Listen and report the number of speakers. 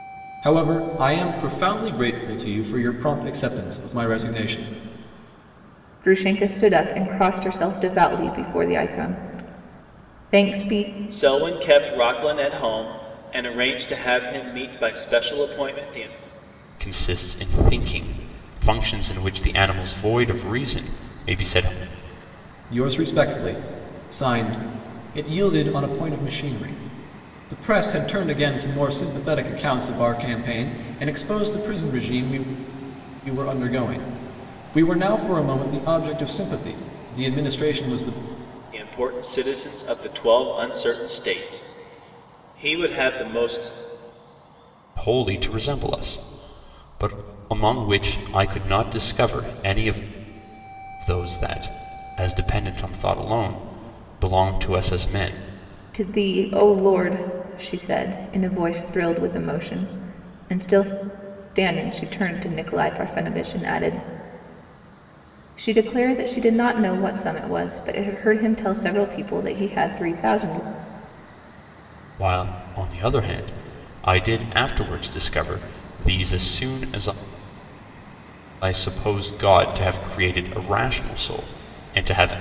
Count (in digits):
4